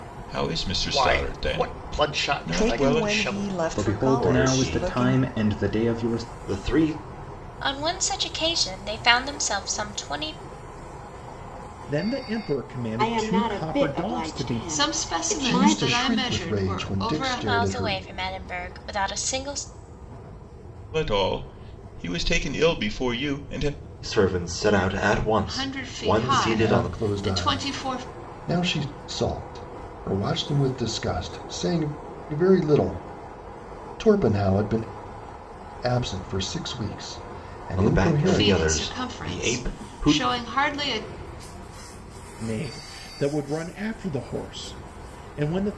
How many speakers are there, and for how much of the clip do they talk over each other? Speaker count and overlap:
10, about 33%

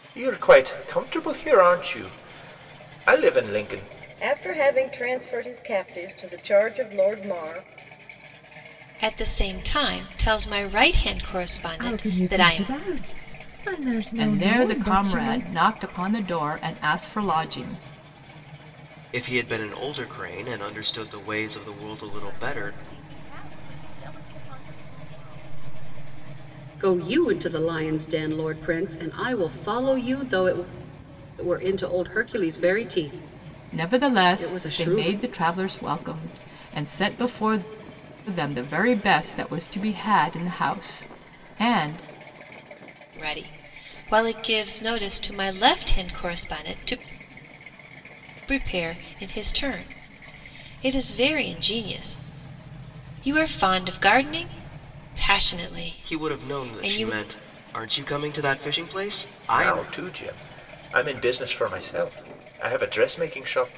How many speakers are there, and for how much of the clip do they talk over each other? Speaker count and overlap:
8, about 9%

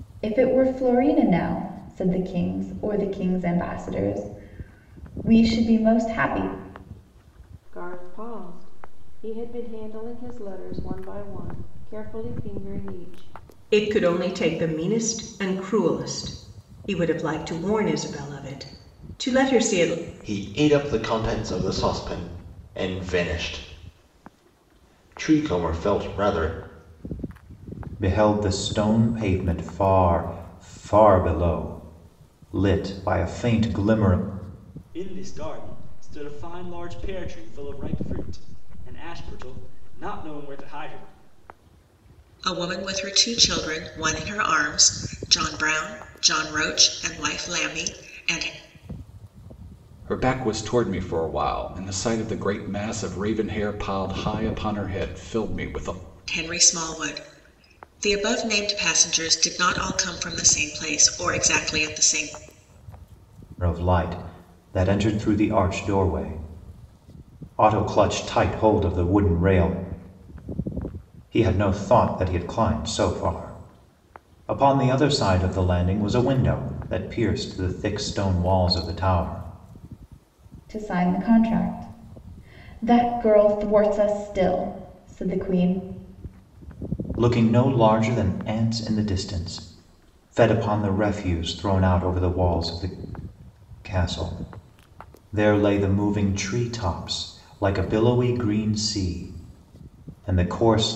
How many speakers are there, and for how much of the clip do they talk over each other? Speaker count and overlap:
8, no overlap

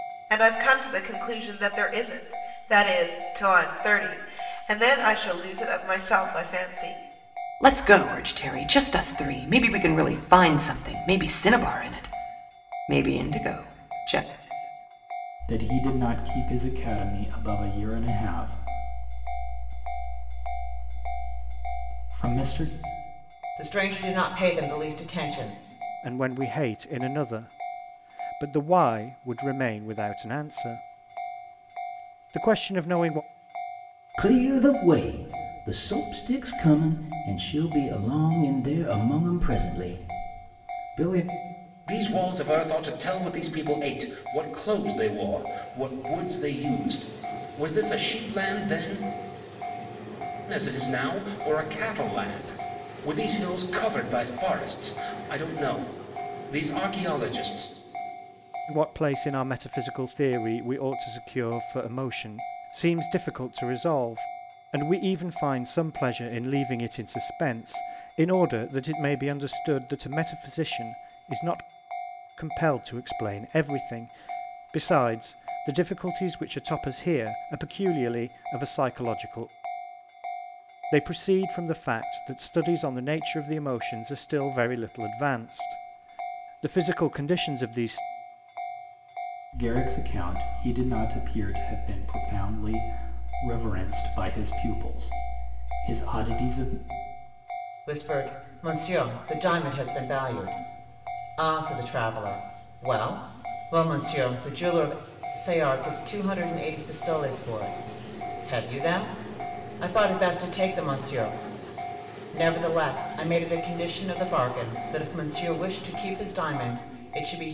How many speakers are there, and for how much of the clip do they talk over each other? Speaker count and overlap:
7, no overlap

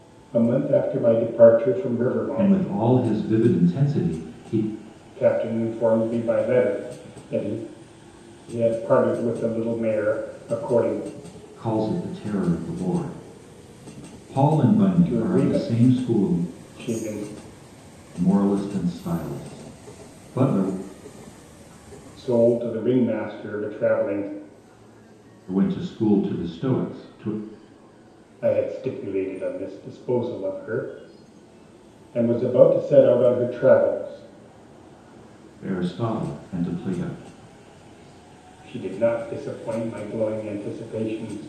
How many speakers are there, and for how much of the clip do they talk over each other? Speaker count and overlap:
2, about 4%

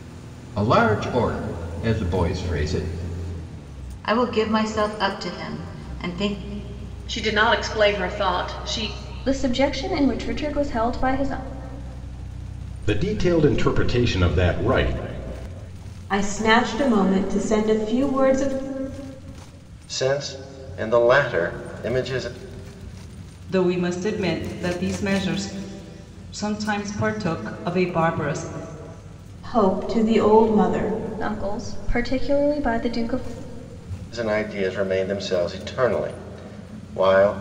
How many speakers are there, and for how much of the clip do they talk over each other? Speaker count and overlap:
8, no overlap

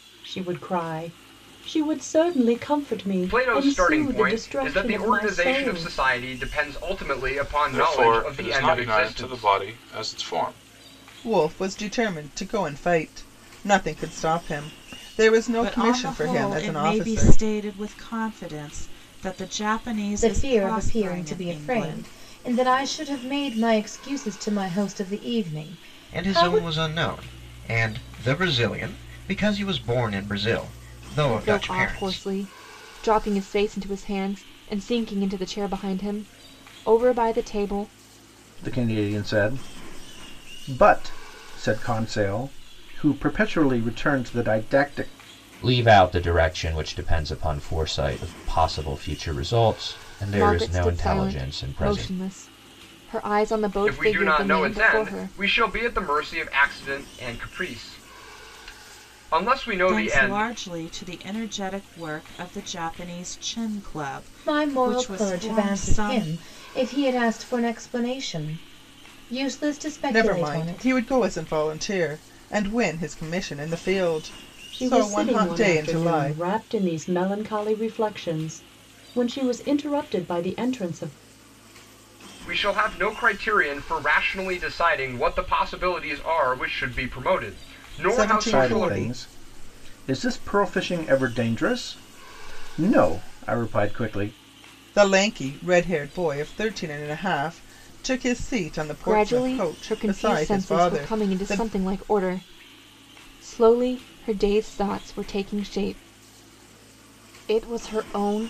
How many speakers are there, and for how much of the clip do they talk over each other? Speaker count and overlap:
10, about 21%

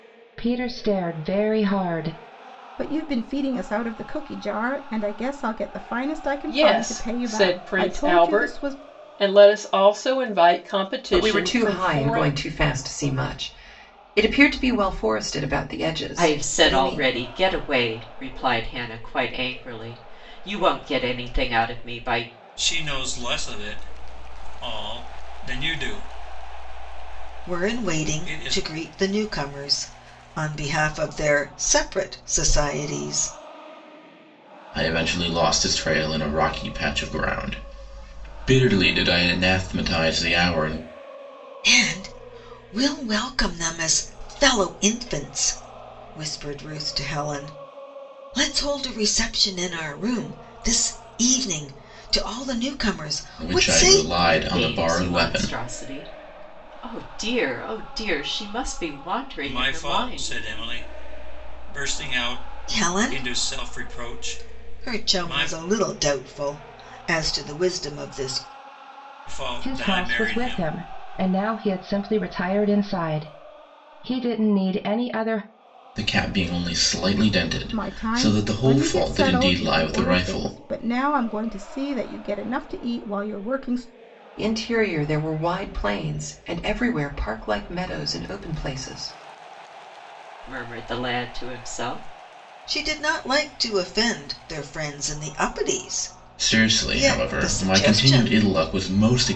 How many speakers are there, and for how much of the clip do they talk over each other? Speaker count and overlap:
8, about 18%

